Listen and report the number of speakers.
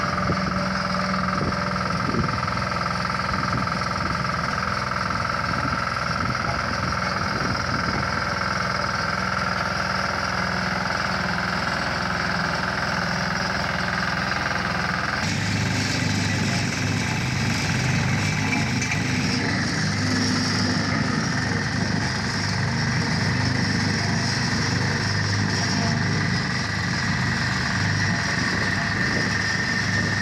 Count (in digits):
0